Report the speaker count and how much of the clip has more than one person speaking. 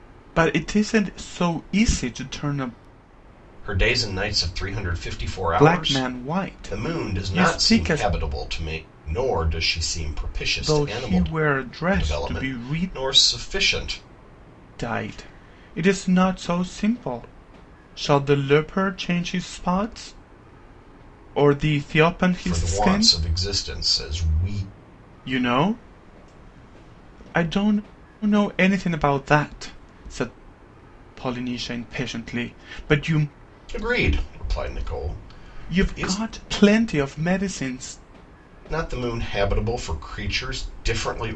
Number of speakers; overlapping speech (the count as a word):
two, about 12%